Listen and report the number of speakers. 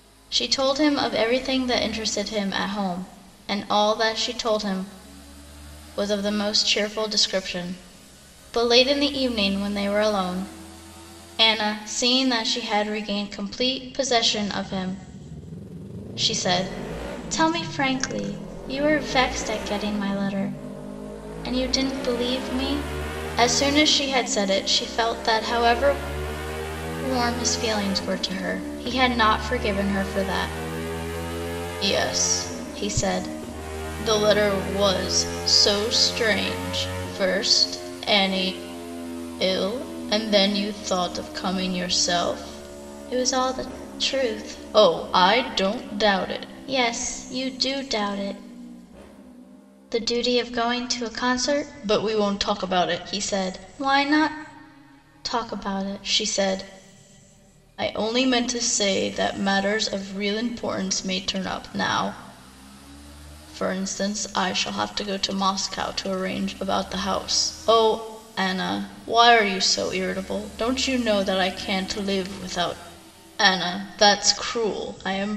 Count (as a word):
one